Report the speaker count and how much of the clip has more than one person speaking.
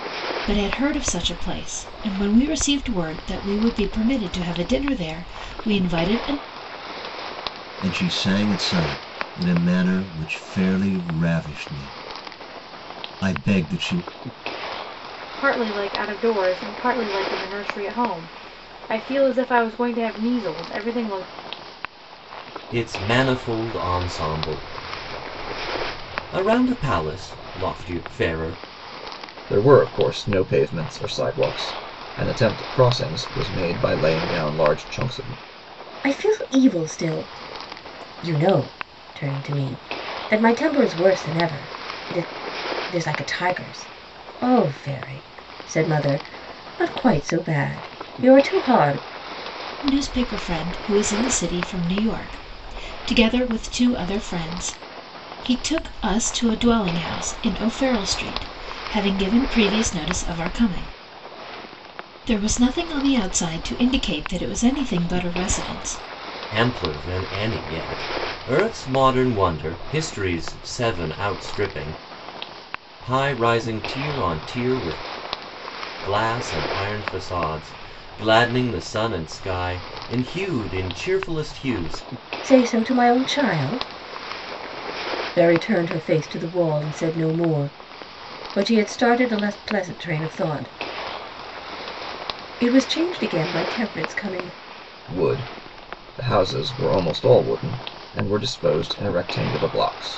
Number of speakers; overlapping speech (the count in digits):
6, no overlap